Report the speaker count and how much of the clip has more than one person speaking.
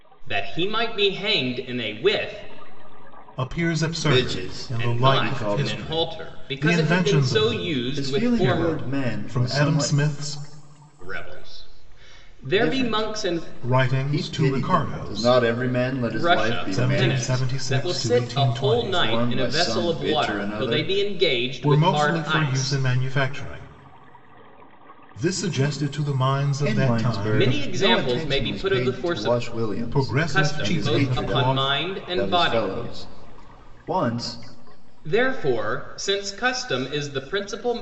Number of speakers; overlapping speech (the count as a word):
three, about 52%